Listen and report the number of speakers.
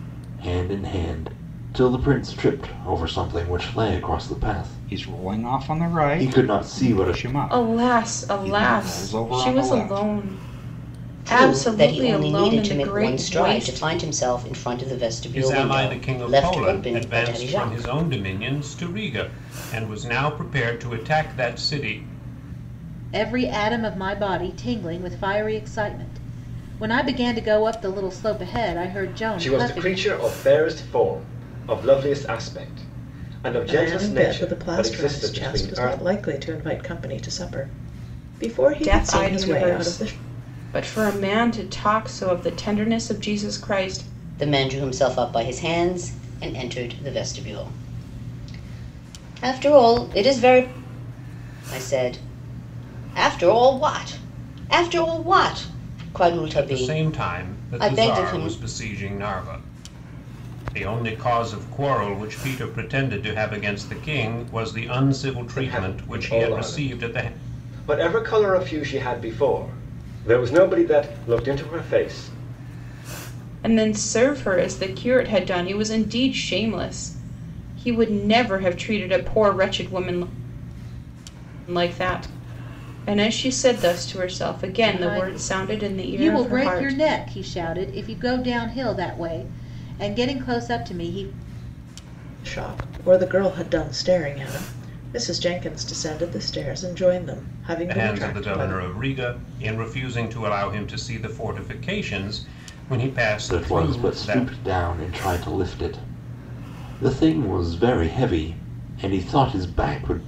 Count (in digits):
8